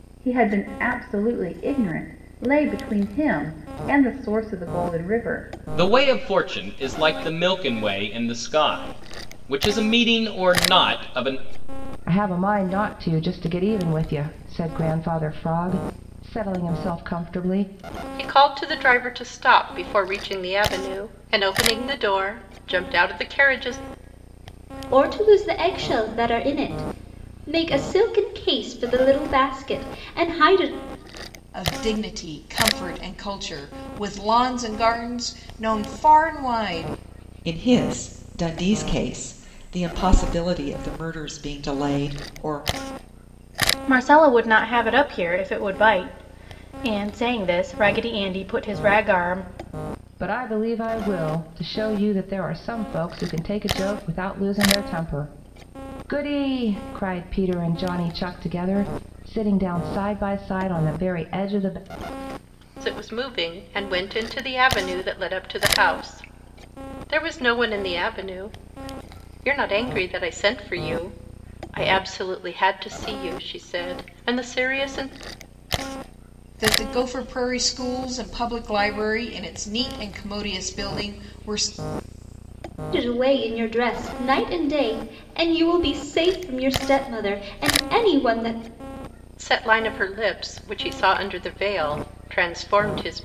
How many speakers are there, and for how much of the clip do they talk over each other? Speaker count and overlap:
8, no overlap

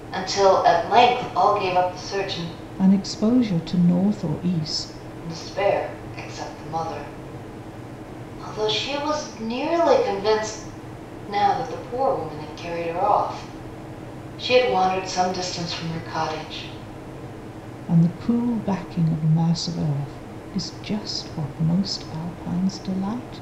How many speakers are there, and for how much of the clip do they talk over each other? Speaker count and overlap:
2, no overlap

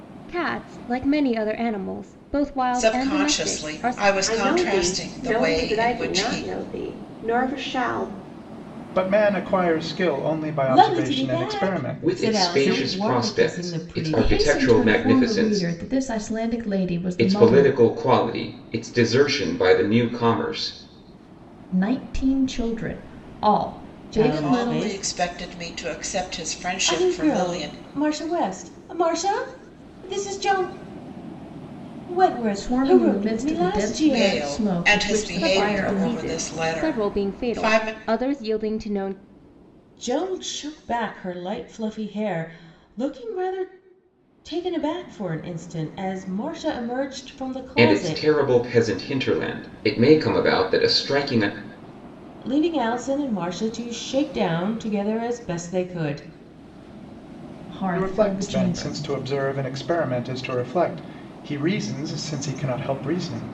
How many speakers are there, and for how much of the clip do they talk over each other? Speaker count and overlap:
7, about 29%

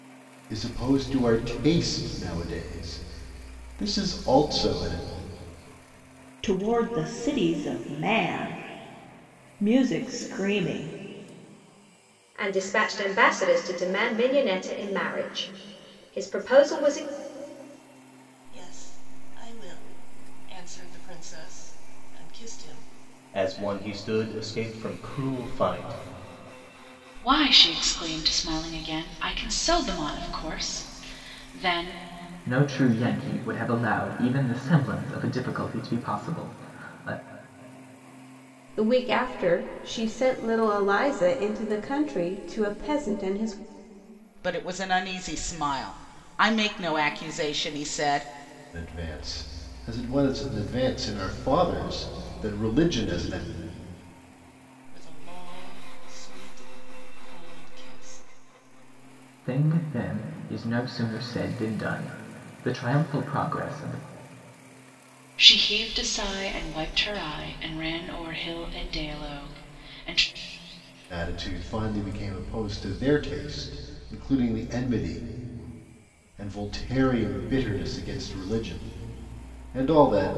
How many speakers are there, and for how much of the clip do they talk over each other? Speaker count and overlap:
9, no overlap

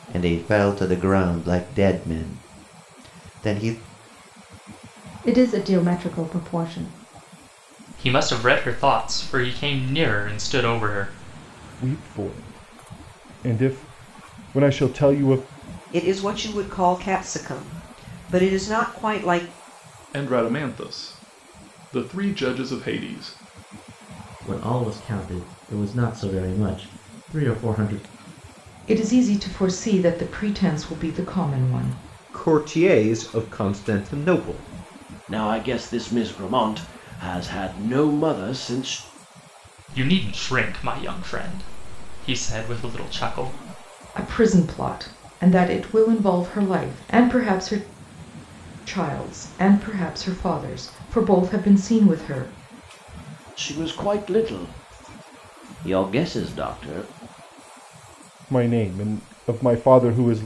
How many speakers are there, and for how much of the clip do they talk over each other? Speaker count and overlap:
10, no overlap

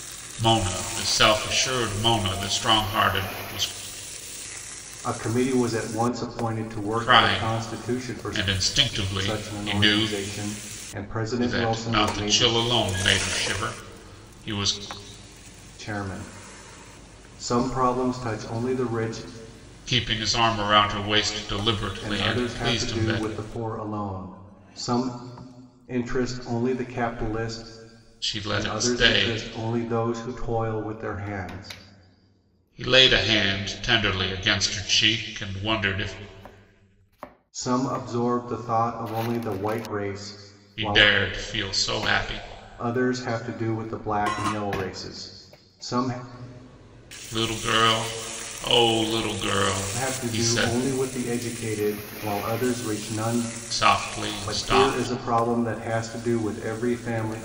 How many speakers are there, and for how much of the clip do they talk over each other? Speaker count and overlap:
2, about 14%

